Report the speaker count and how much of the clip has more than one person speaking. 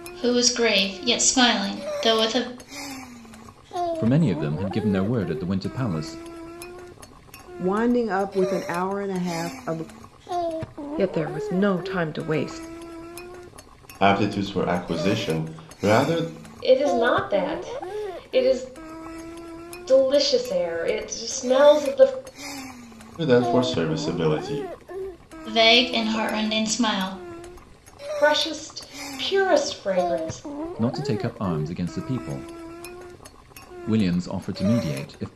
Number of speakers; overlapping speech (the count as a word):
six, no overlap